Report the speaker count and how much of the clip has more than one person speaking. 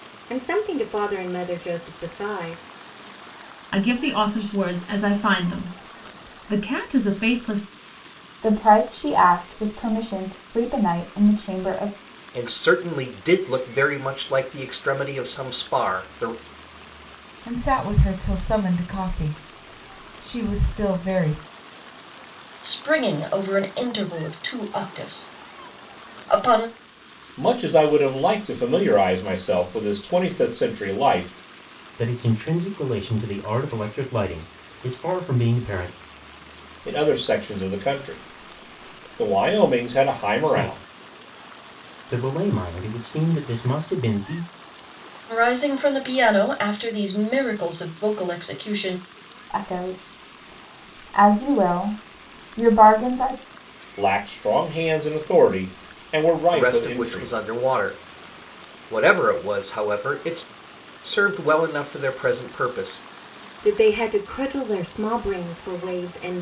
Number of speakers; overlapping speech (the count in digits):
8, about 2%